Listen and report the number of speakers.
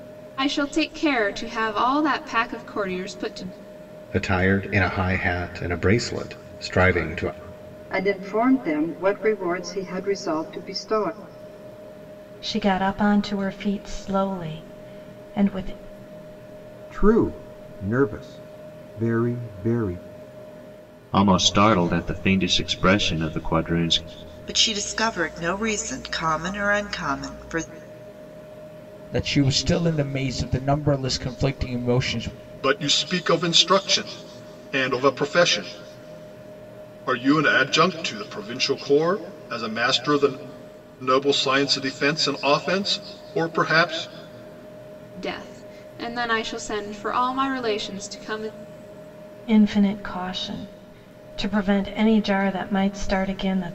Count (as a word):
nine